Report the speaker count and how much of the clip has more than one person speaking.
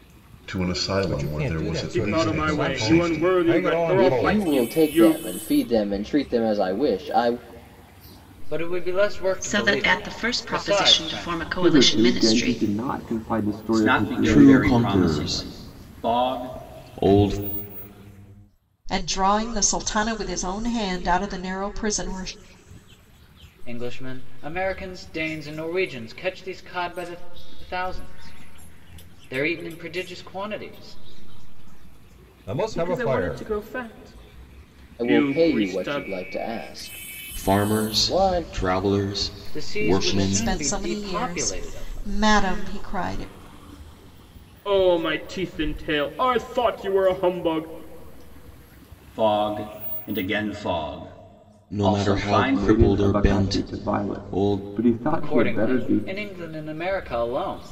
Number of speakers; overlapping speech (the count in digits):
10, about 35%